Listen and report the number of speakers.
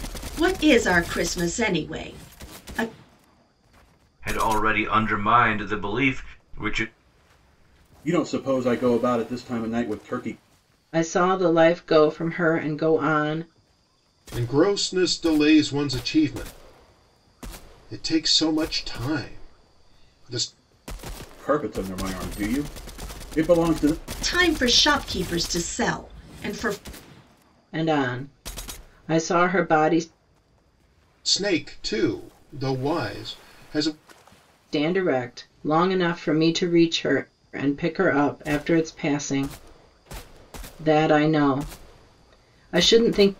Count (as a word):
five